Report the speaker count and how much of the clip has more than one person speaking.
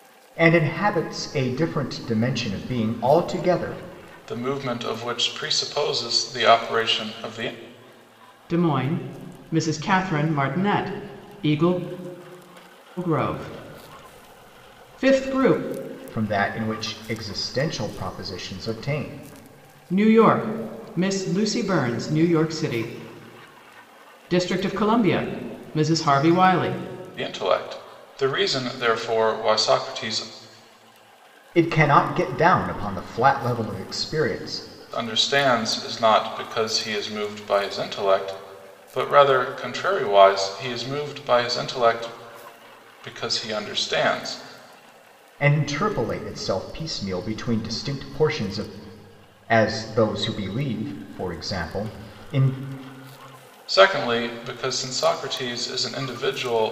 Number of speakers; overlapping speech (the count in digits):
3, no overlap